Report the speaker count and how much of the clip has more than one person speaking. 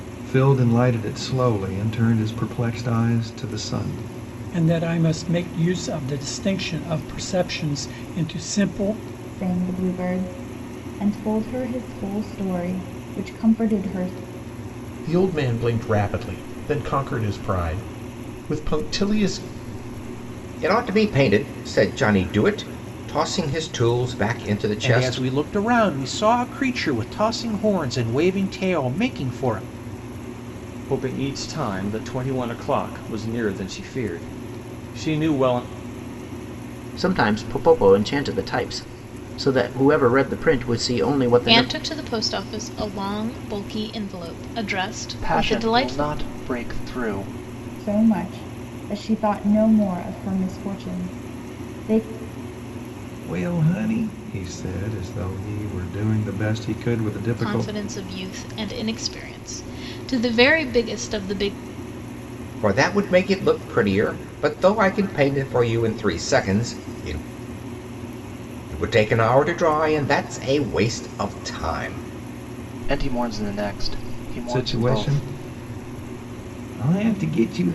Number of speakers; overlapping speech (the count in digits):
10, about 4%